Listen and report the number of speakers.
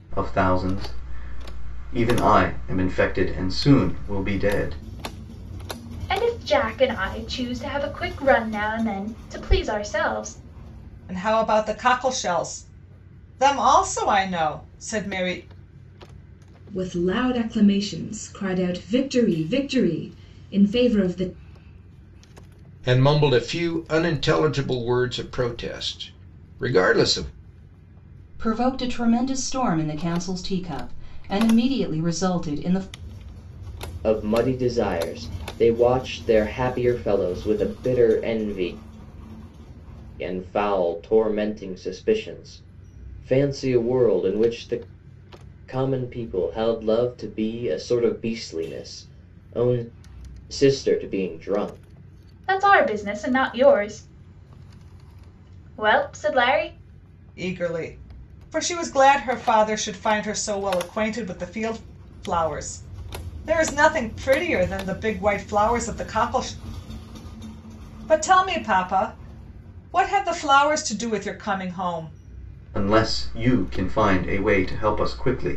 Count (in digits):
7